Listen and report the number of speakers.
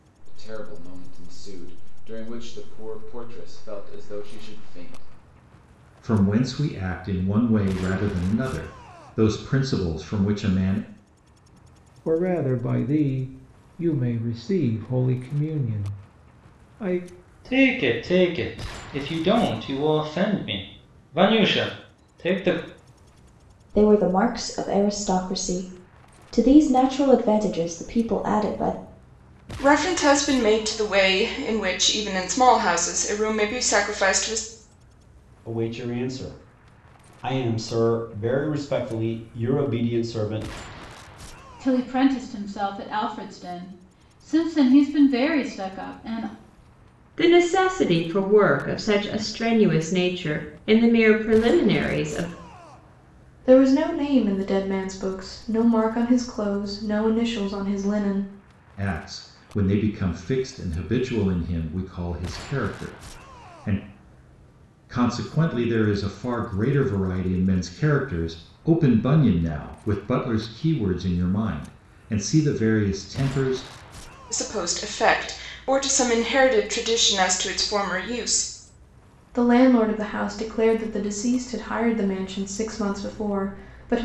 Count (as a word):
ten